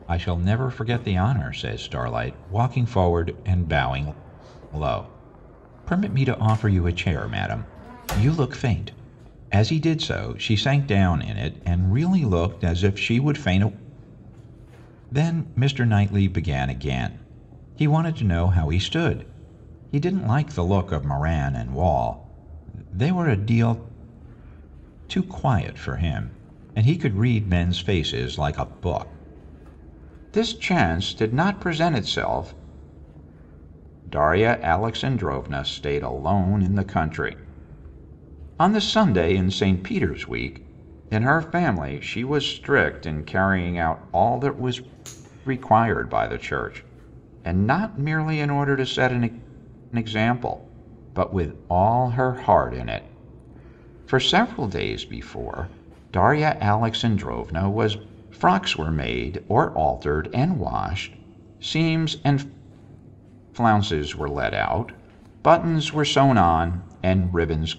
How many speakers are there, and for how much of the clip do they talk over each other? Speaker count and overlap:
1, no overlap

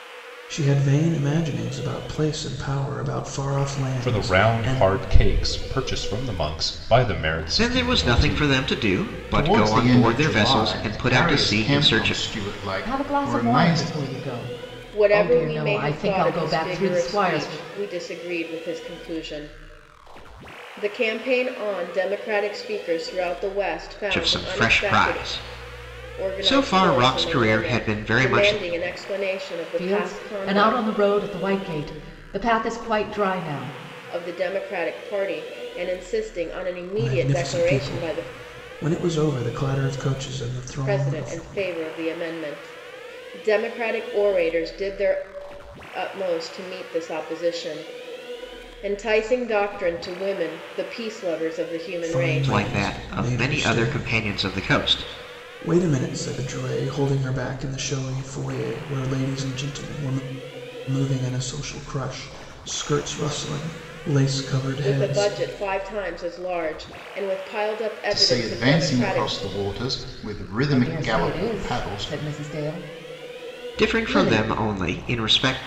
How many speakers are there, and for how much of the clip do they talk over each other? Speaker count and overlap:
6, about 28%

